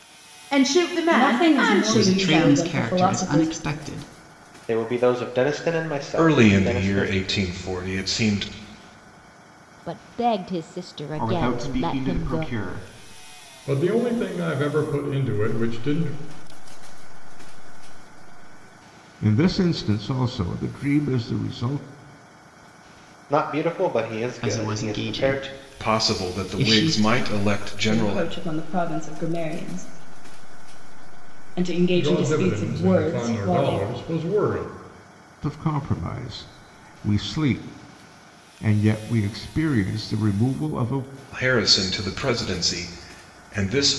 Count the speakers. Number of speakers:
10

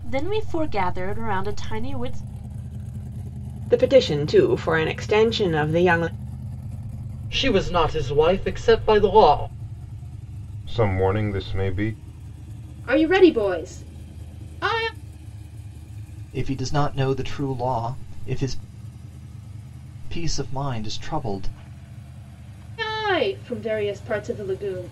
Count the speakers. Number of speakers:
6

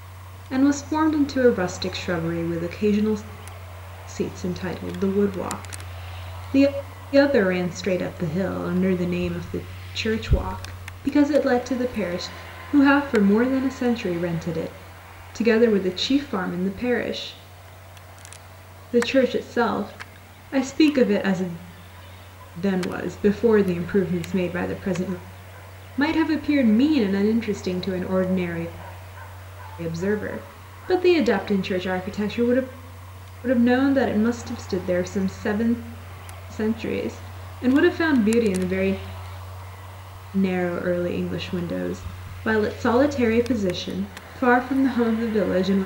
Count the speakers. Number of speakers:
1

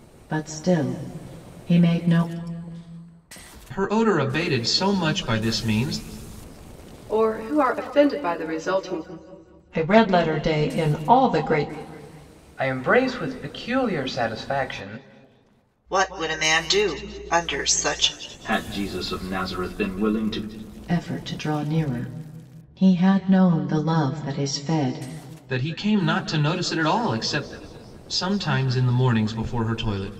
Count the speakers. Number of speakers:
7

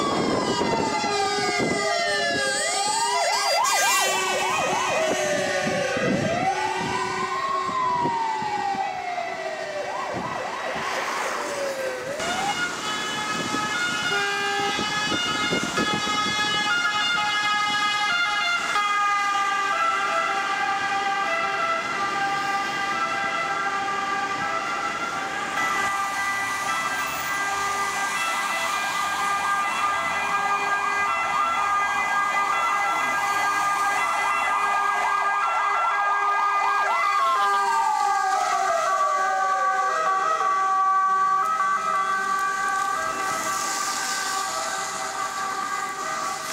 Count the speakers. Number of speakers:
0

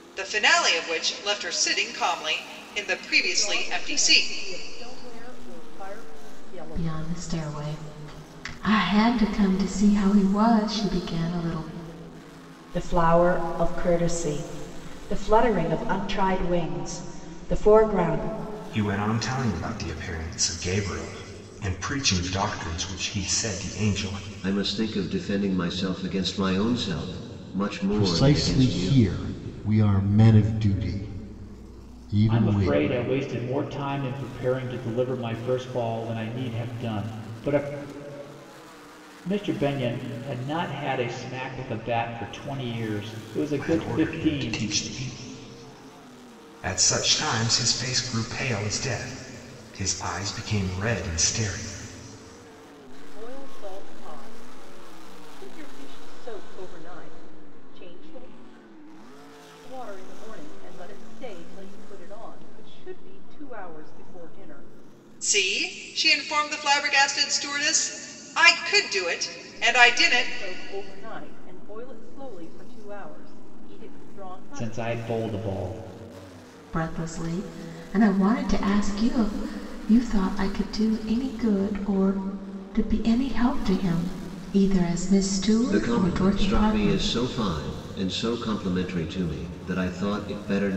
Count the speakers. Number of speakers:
8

